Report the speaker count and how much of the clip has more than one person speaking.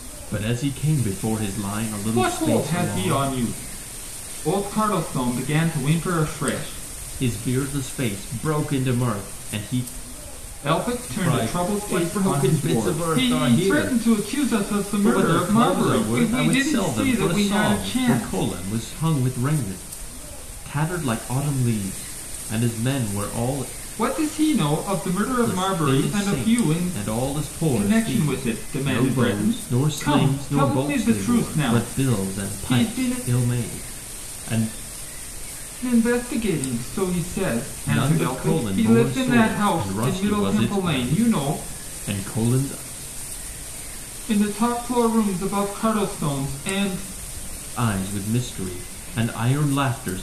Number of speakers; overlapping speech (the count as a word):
two, about 36%